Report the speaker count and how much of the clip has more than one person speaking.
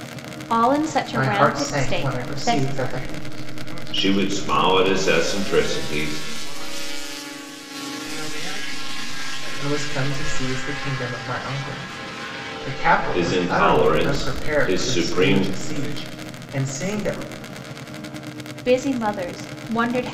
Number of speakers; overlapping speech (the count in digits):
4, about 40%